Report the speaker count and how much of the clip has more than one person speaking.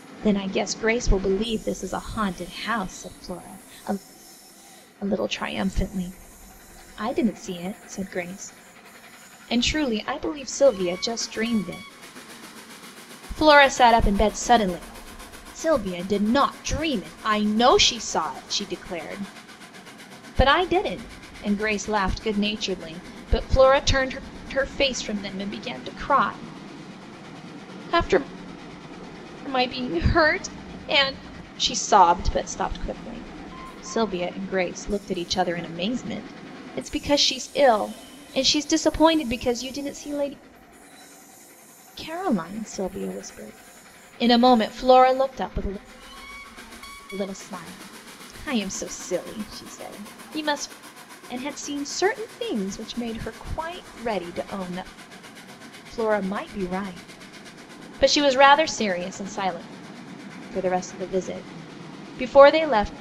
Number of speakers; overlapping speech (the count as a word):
one, no overlap